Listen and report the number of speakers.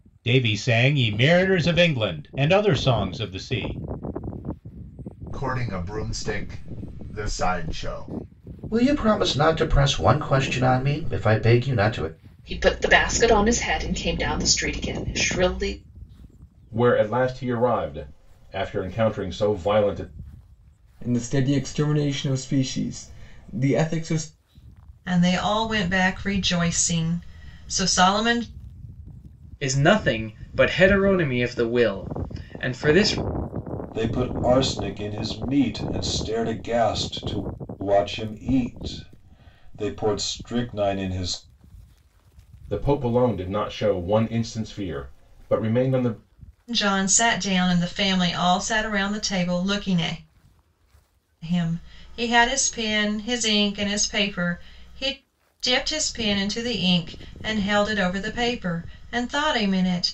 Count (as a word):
nine